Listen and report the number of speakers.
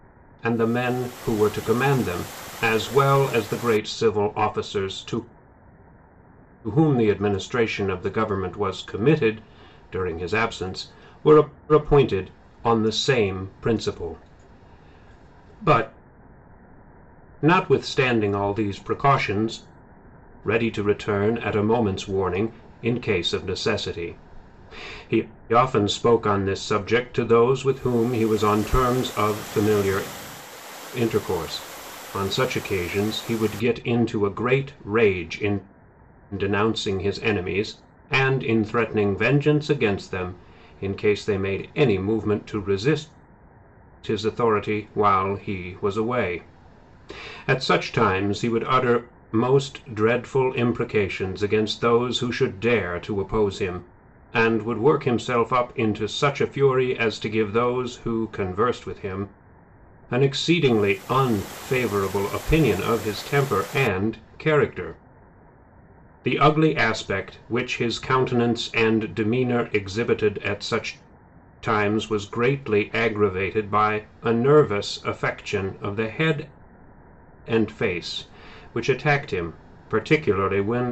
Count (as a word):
one